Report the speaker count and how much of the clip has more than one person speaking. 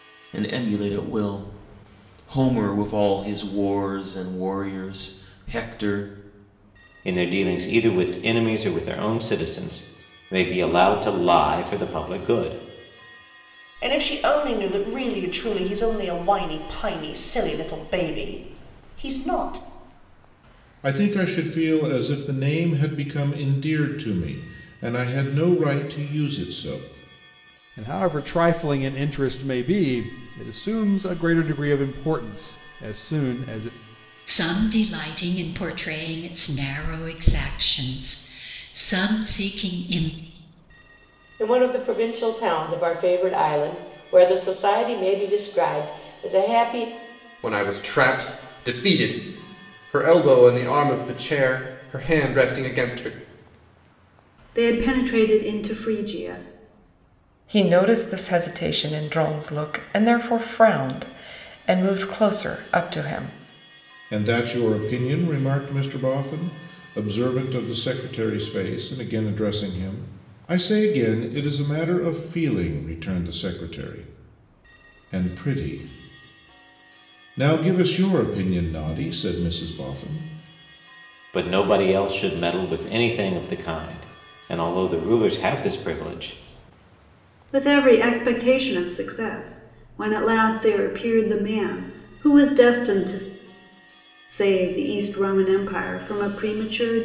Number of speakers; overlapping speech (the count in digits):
10, no overlap